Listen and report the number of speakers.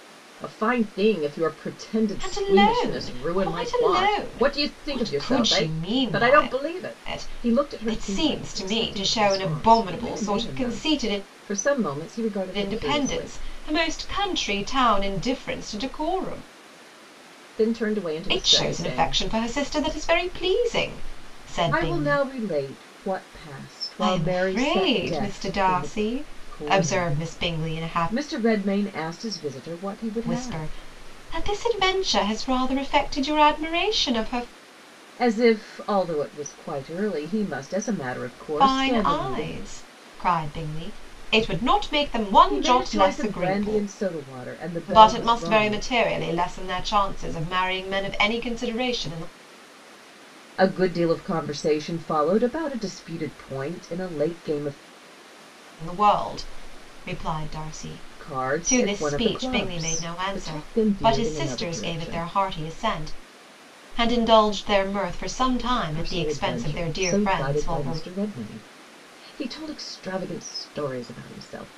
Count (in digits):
2